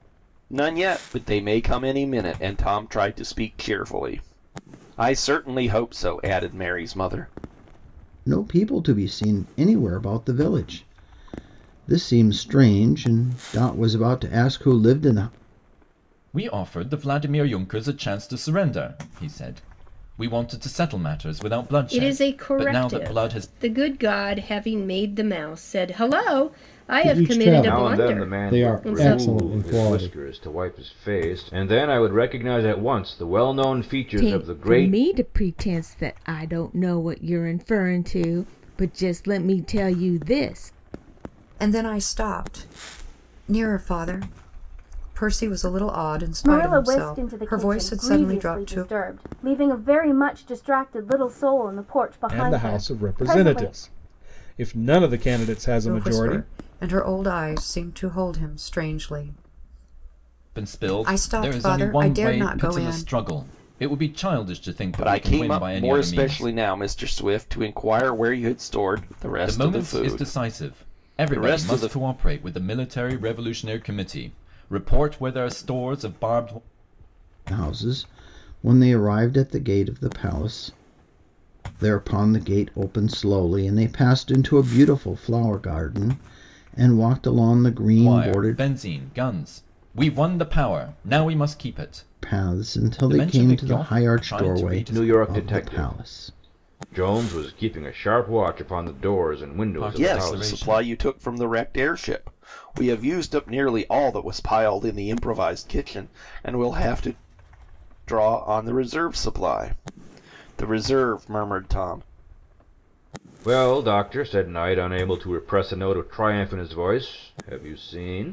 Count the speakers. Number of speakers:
ten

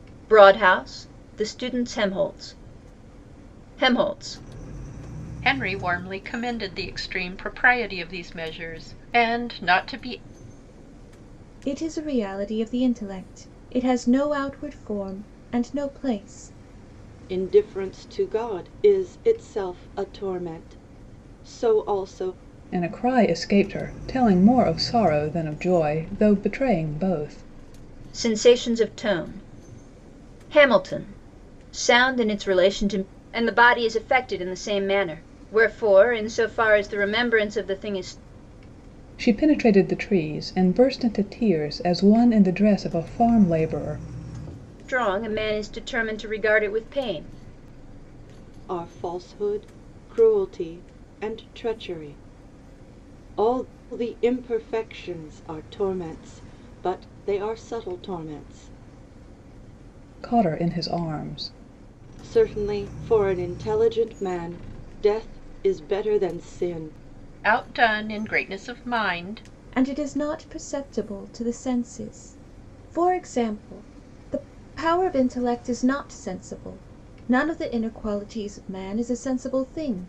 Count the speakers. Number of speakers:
five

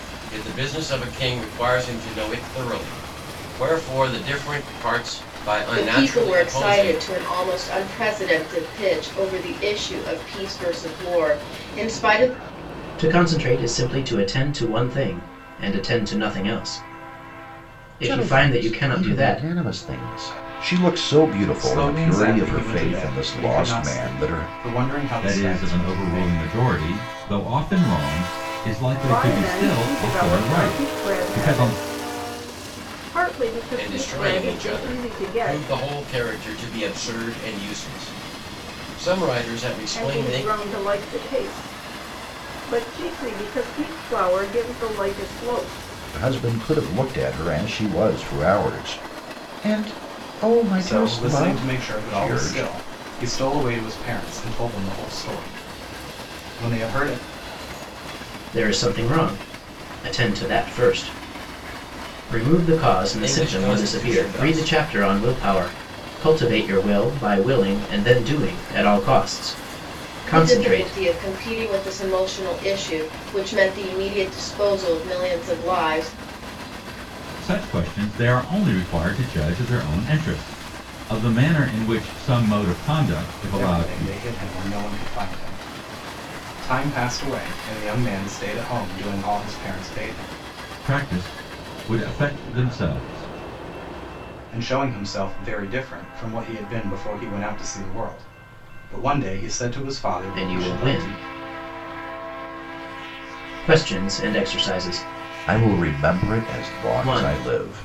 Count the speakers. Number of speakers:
seven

